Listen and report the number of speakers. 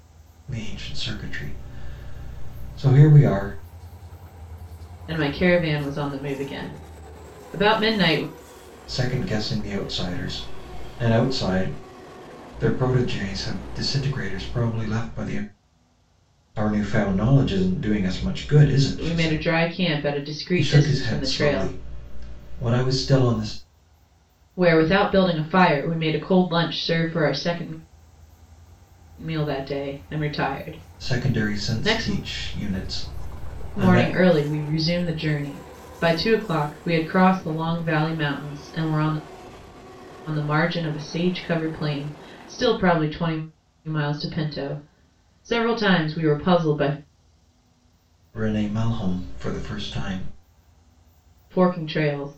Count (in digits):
2